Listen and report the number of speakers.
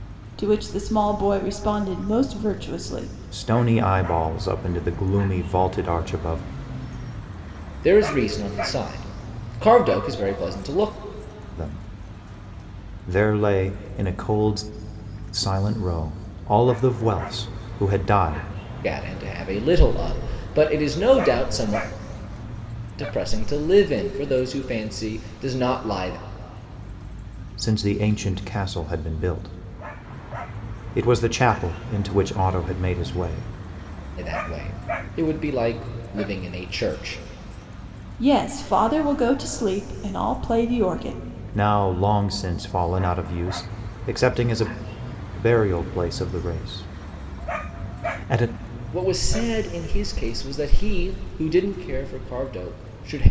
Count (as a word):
three